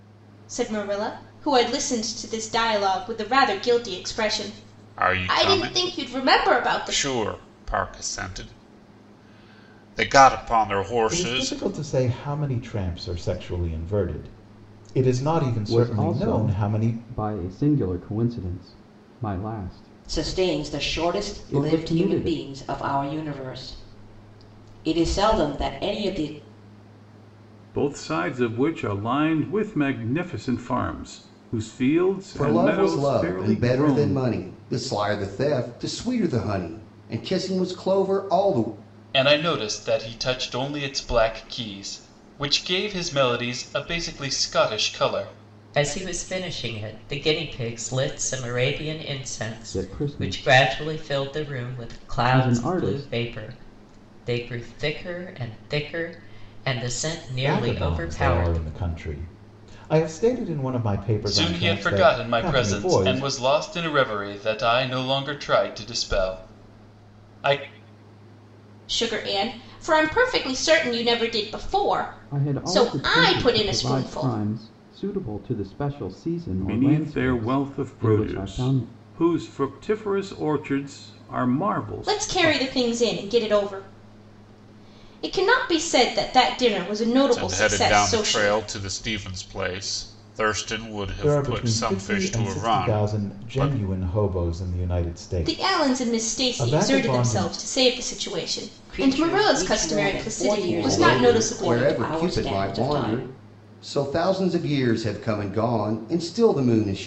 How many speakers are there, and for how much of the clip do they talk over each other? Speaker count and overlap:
9, about 29%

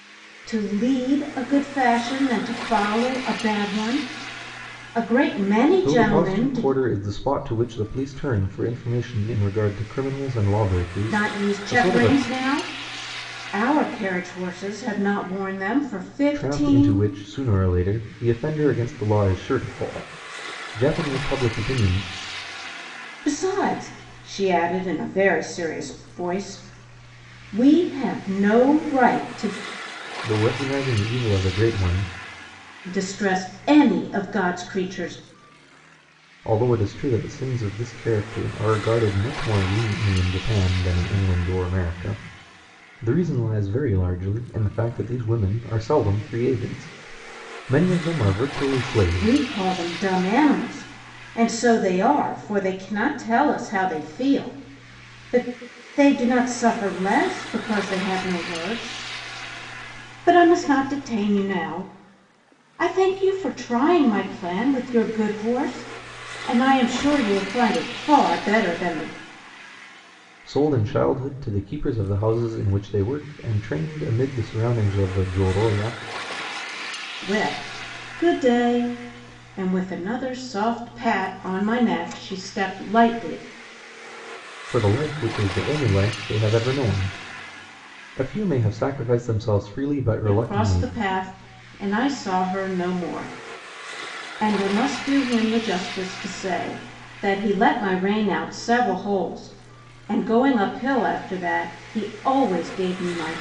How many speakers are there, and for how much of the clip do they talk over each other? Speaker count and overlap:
2, about 4%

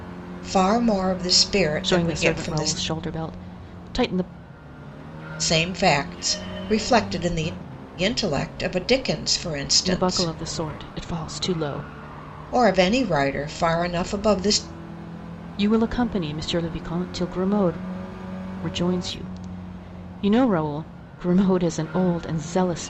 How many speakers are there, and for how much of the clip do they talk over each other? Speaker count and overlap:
2, about 6%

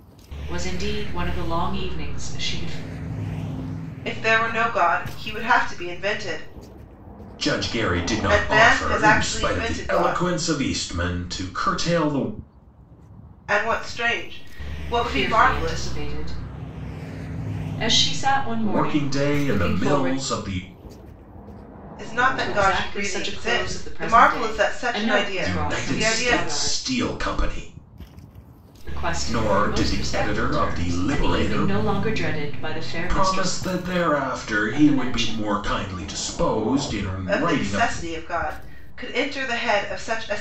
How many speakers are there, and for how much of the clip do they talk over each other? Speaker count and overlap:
3, about 32%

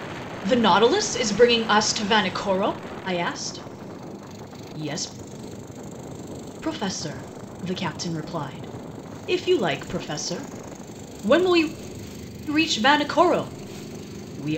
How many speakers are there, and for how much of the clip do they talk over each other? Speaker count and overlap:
1, no overlap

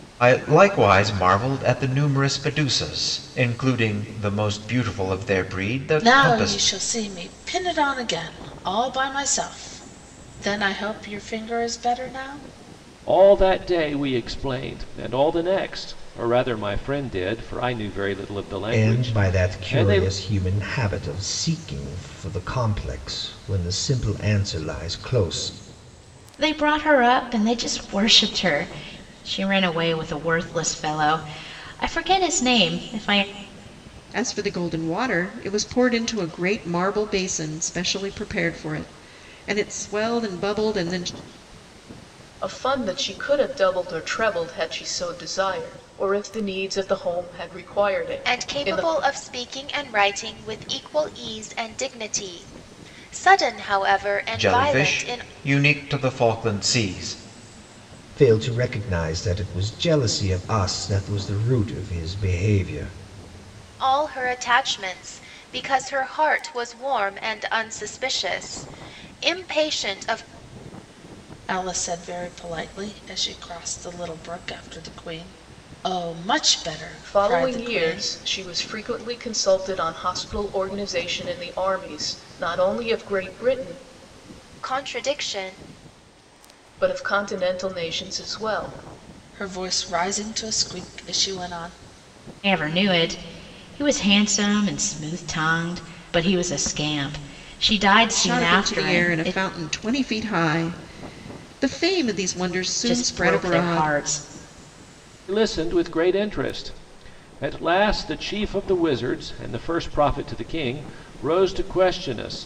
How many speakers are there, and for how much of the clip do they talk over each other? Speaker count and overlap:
8, about 6%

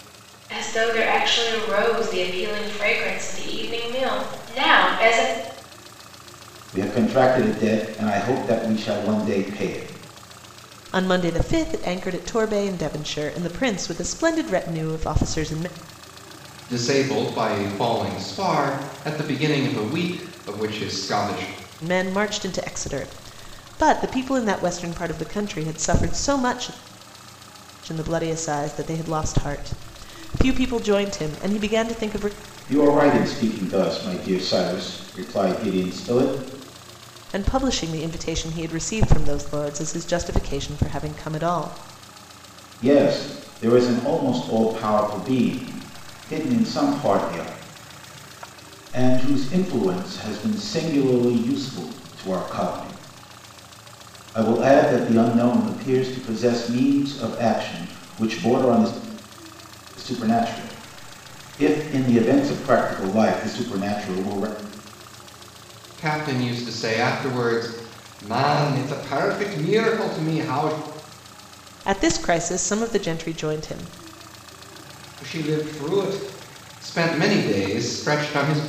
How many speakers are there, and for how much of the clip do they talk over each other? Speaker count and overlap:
4, no overlap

